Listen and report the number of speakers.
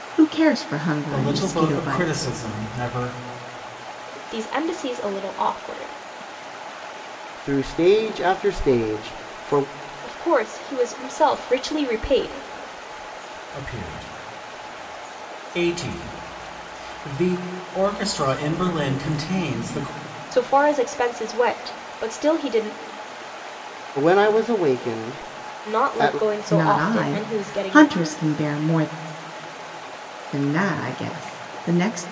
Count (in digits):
4